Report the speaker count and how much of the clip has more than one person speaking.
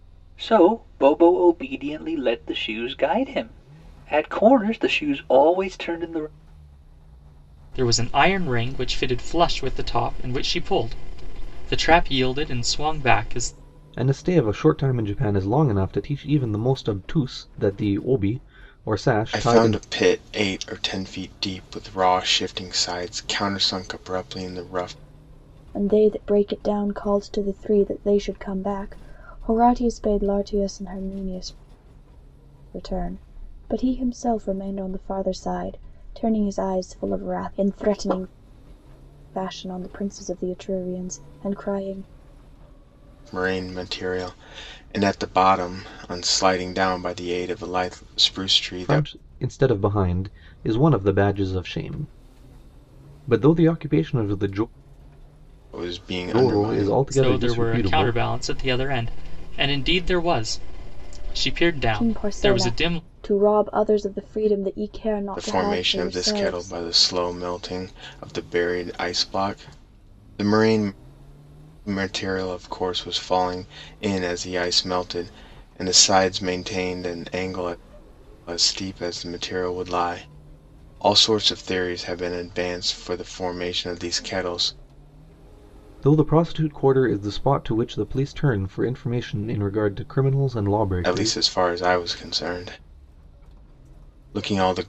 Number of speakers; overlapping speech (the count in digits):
5, about 6%